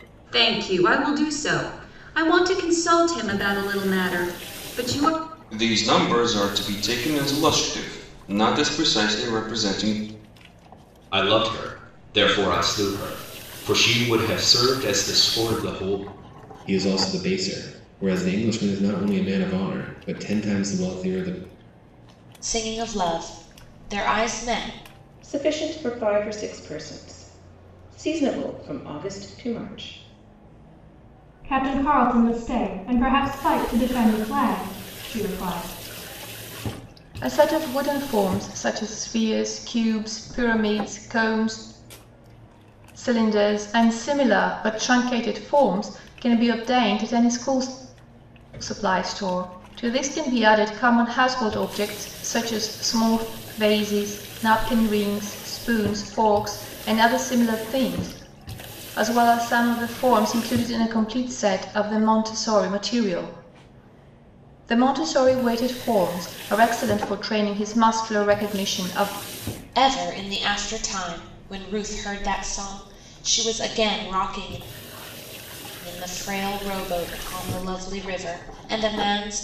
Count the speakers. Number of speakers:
eight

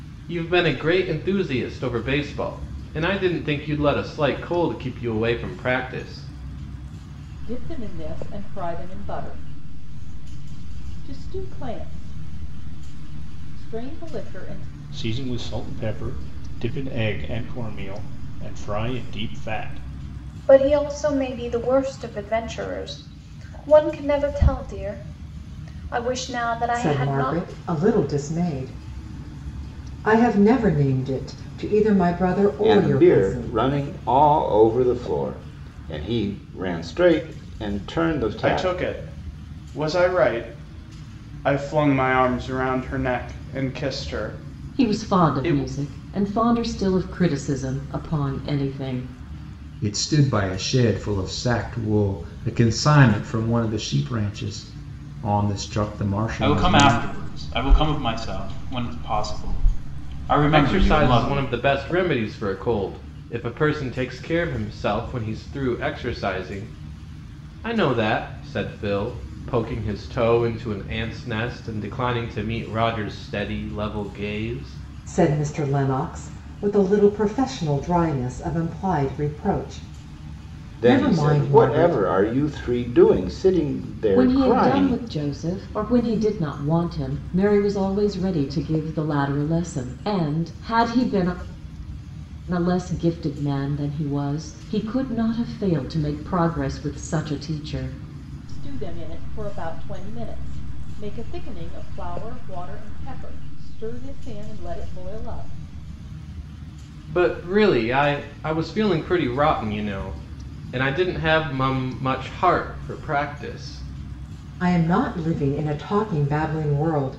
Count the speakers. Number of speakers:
ten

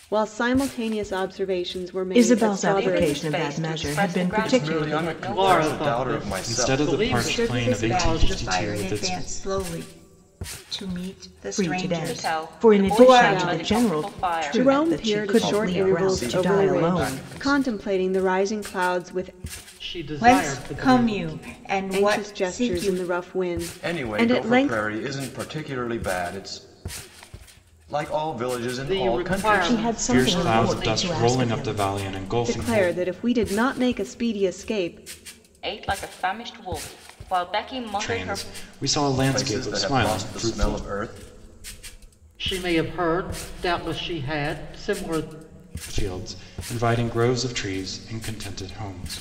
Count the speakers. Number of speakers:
seven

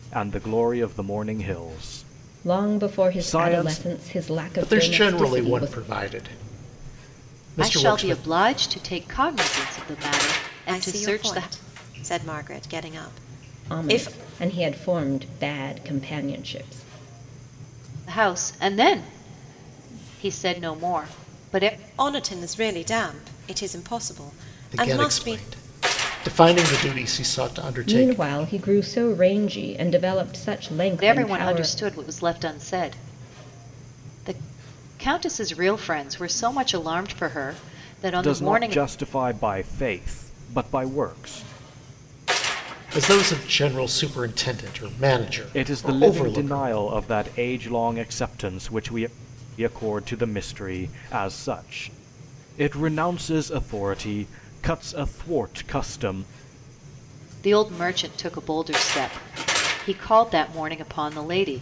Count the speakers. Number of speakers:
five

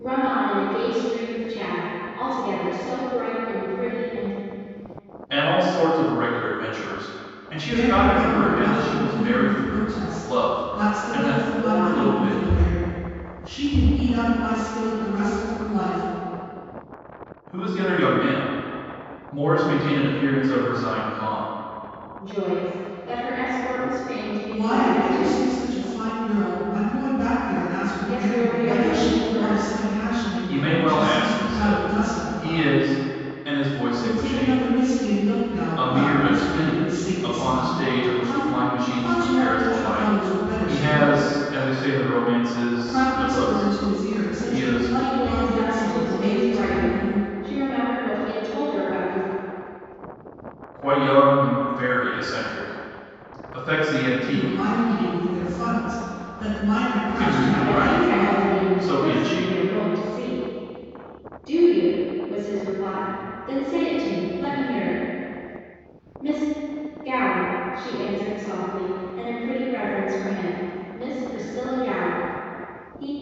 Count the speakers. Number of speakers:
three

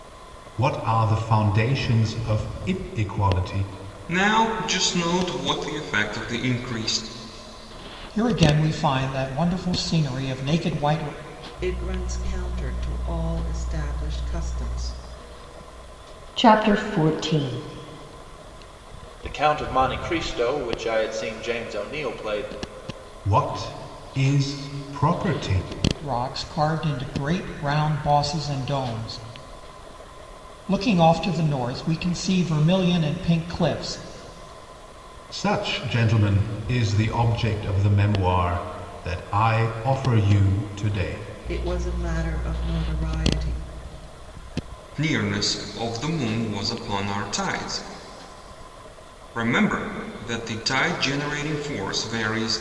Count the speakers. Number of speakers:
six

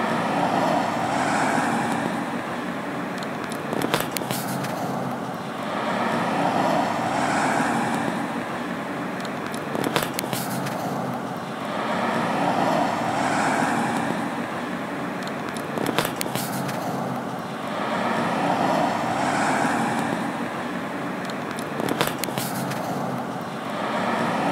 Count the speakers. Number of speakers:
zero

